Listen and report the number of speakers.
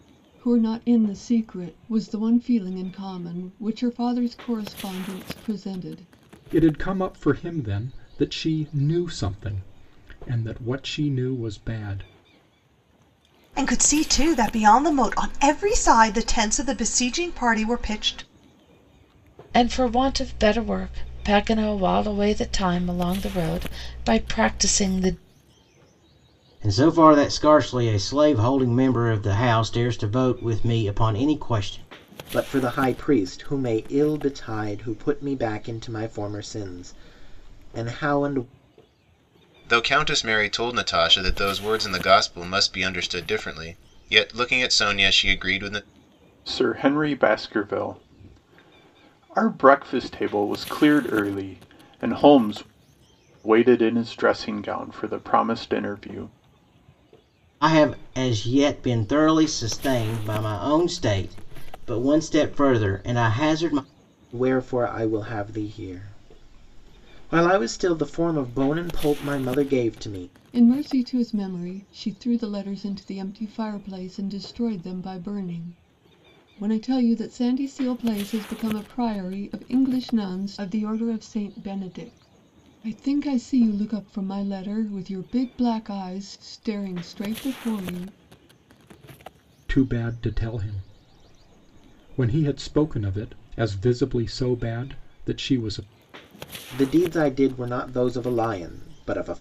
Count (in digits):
8